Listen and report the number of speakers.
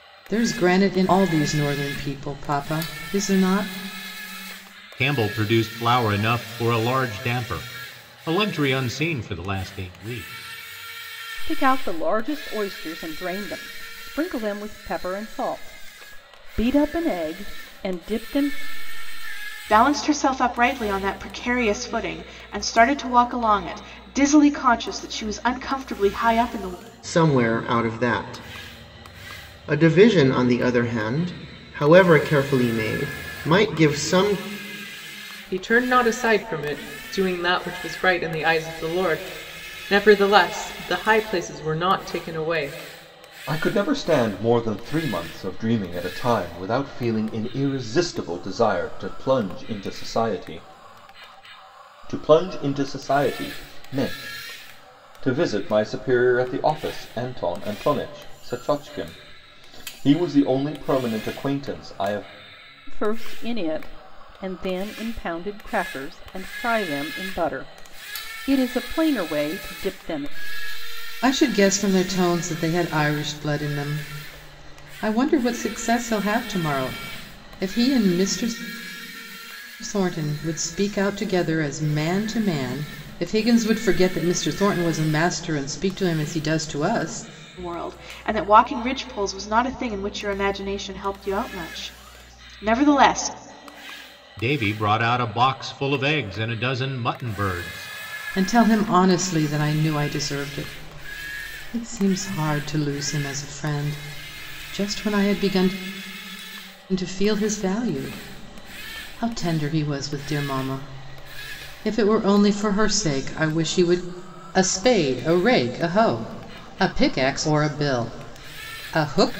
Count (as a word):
seven